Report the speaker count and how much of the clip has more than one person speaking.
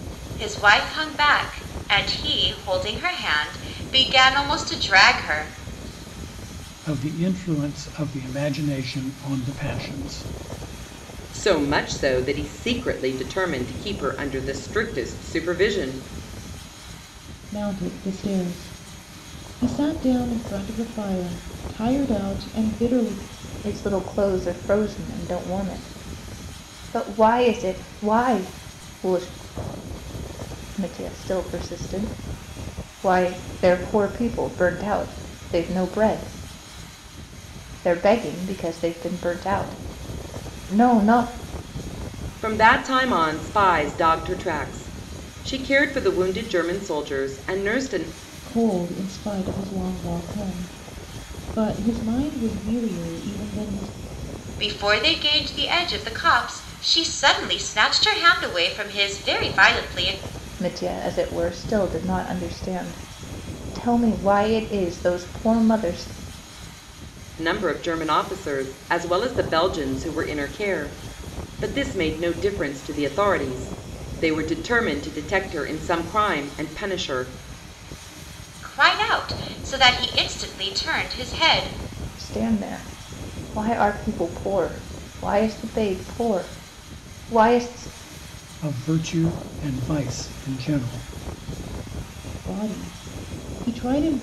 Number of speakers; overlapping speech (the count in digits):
5, no overlap